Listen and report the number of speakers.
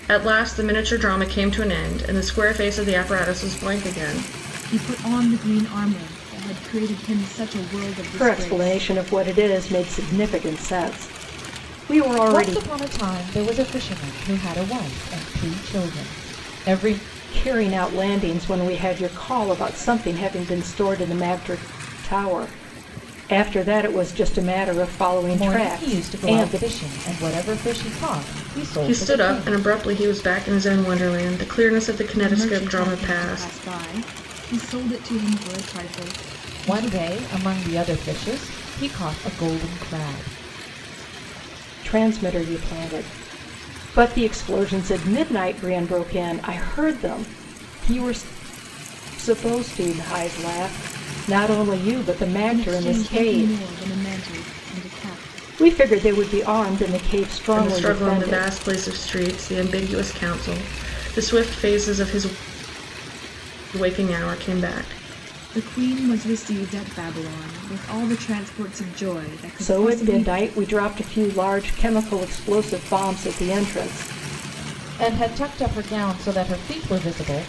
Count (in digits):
4